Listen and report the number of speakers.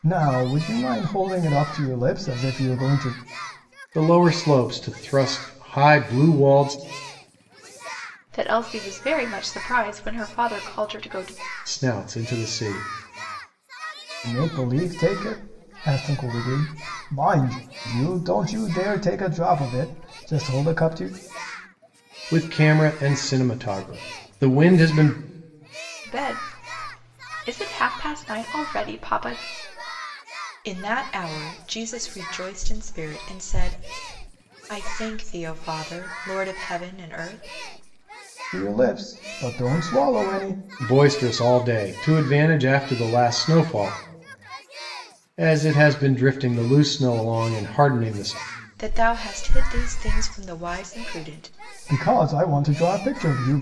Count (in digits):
3